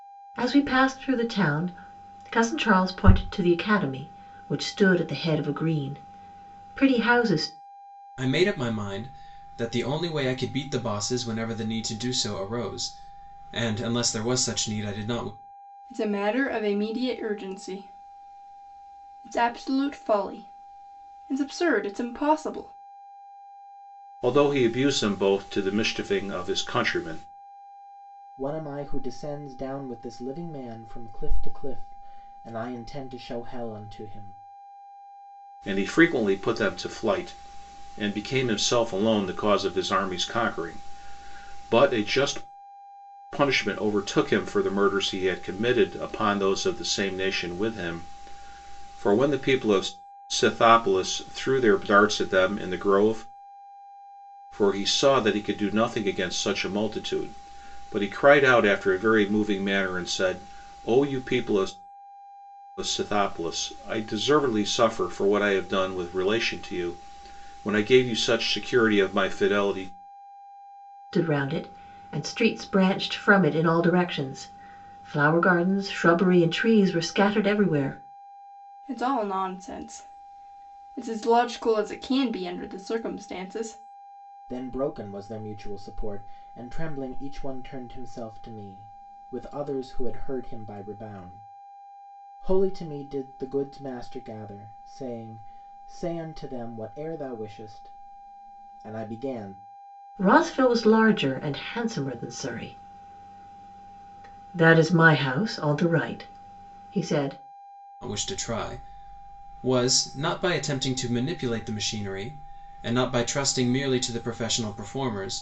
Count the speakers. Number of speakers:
5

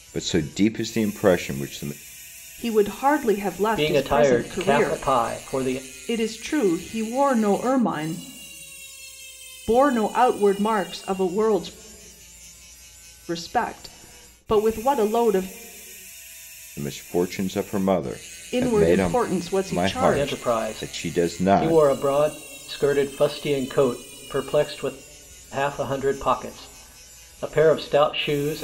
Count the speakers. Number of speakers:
3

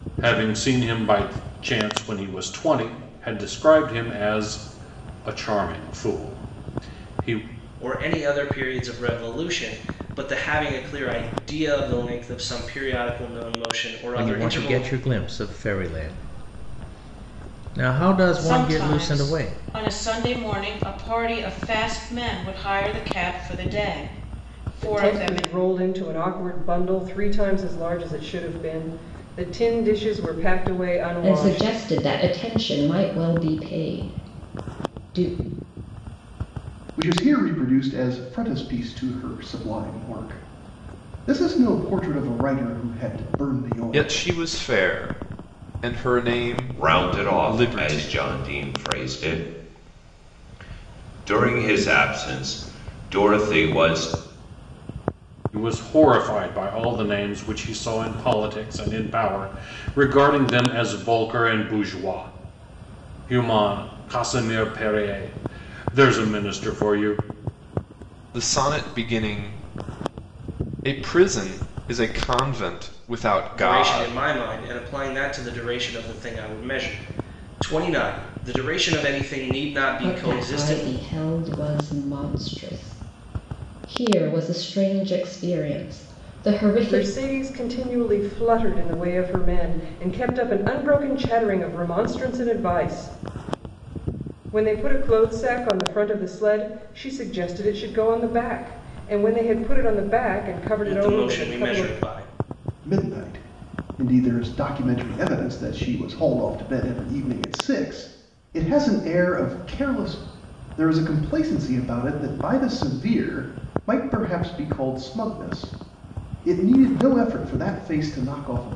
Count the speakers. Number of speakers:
9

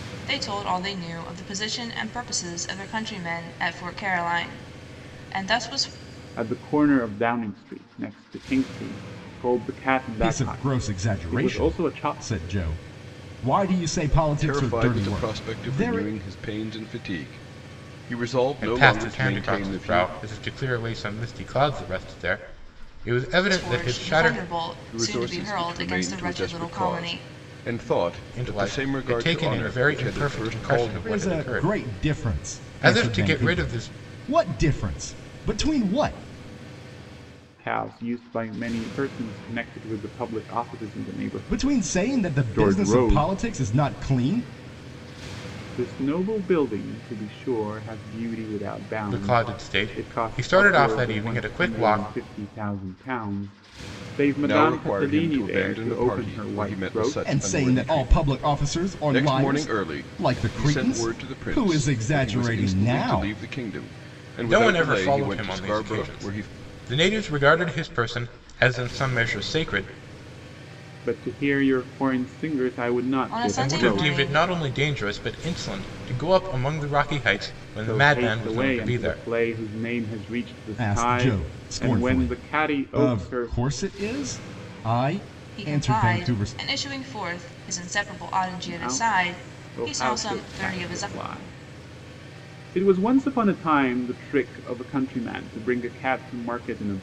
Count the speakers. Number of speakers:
5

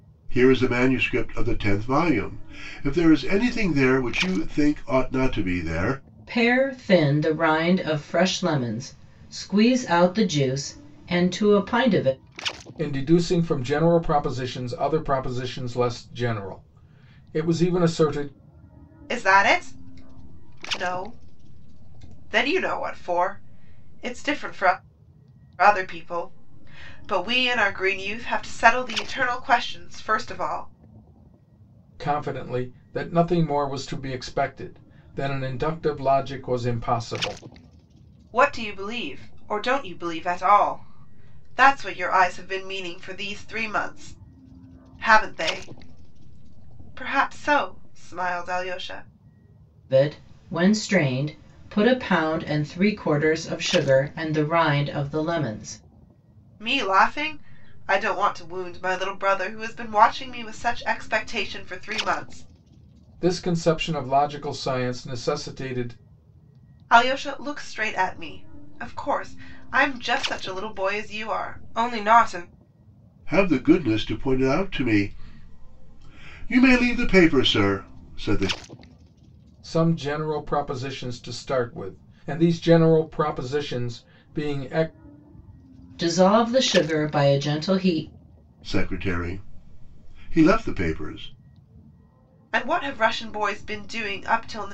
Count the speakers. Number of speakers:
4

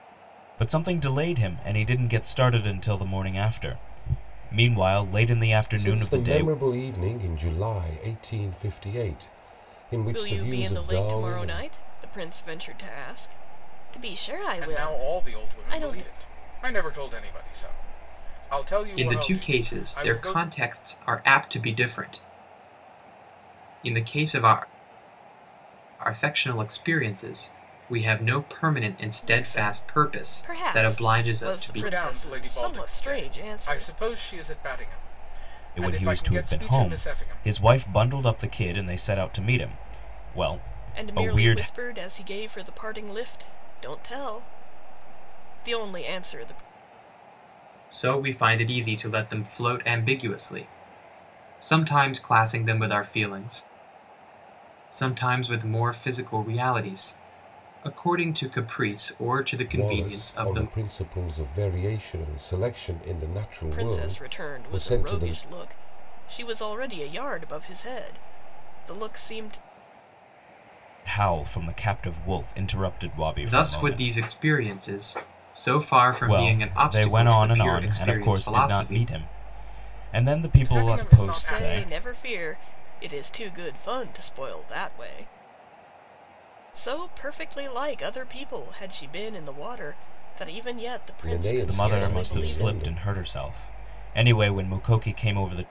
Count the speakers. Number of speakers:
5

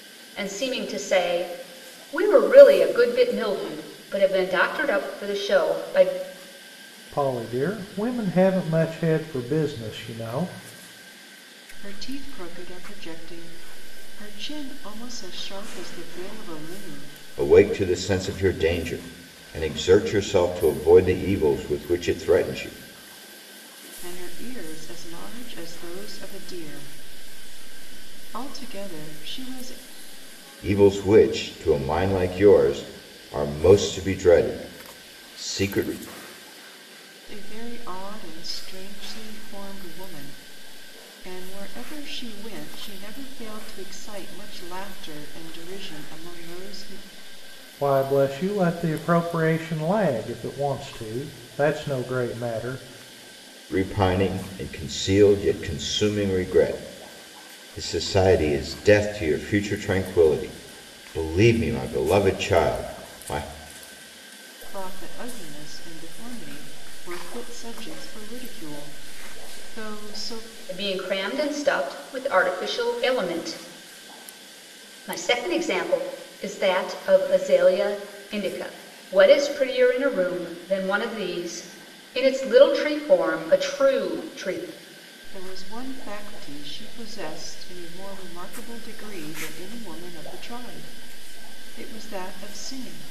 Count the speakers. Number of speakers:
4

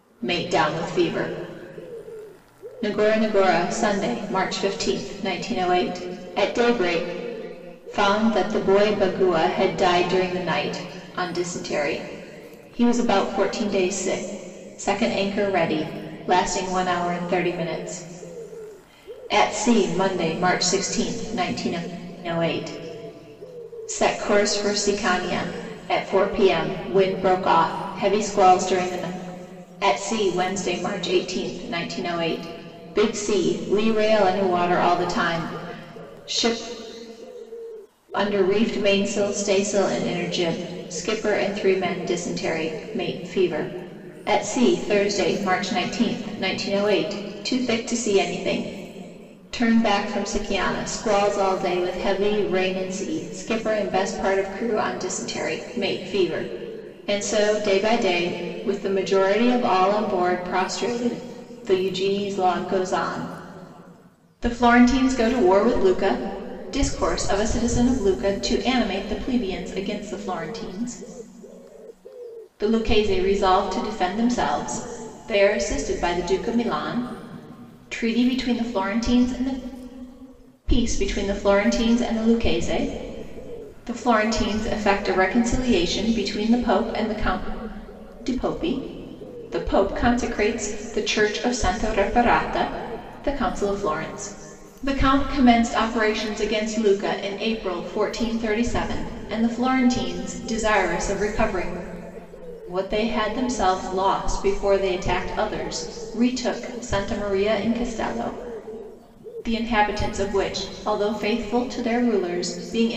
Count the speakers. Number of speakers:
1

